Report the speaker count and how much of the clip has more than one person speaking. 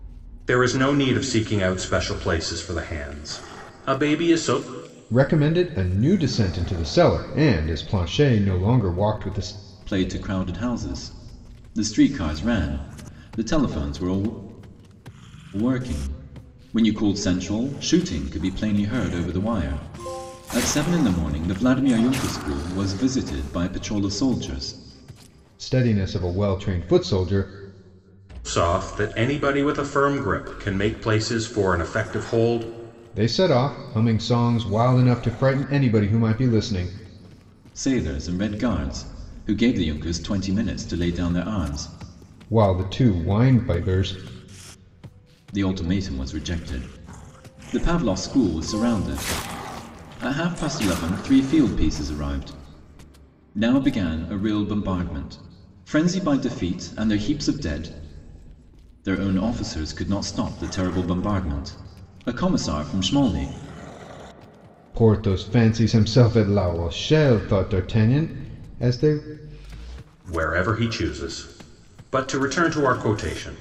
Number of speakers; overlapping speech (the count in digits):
3, no overlap